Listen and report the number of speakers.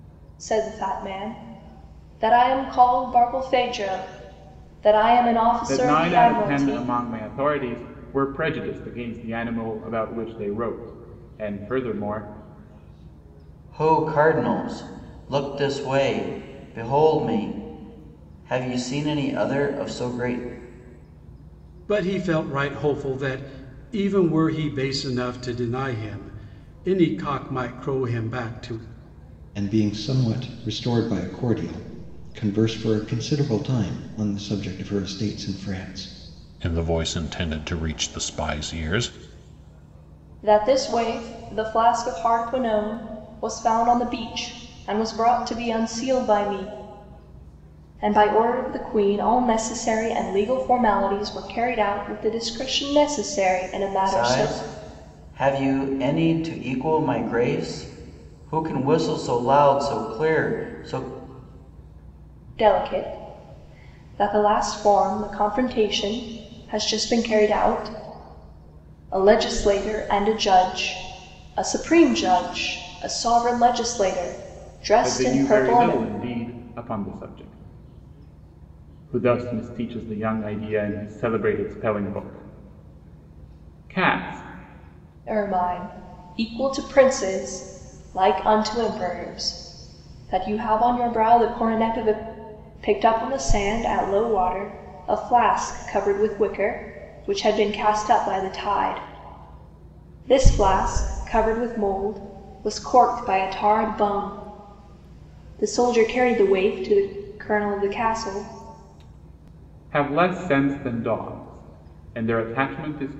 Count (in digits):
6